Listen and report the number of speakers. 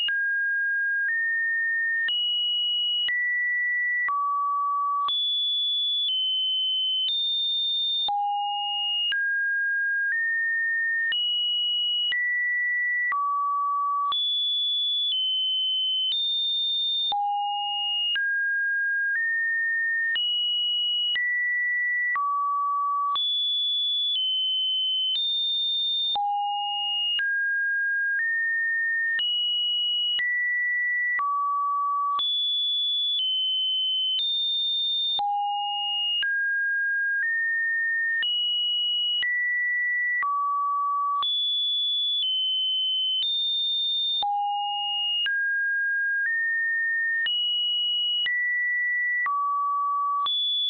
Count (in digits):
0